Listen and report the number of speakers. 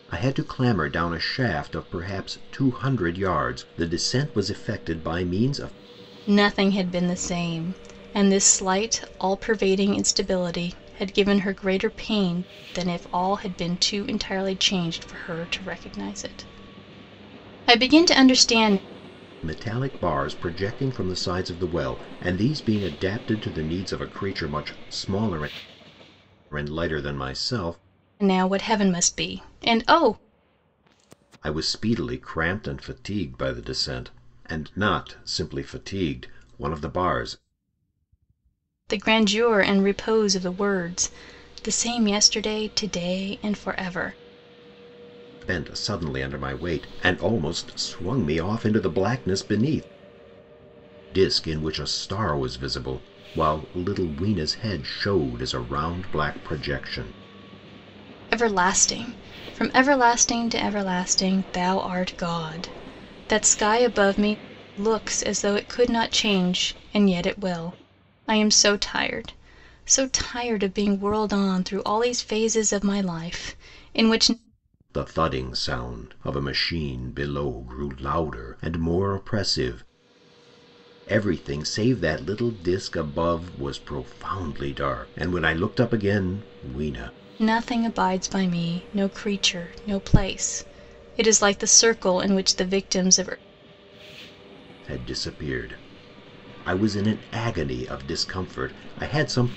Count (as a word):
two